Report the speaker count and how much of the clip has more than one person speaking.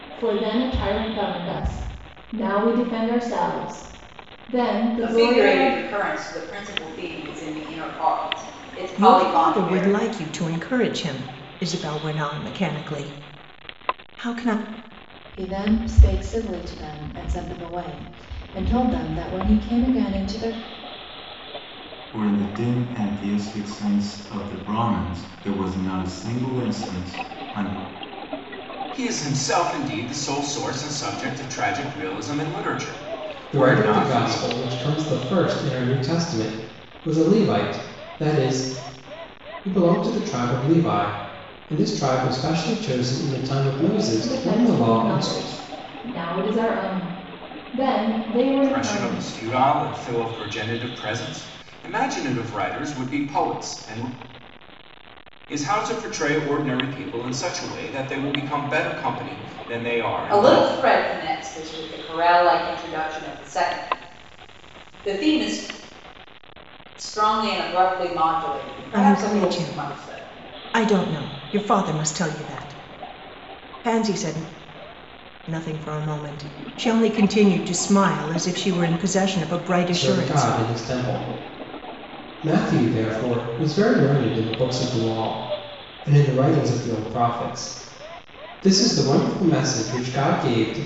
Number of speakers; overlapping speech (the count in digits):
7, about 8%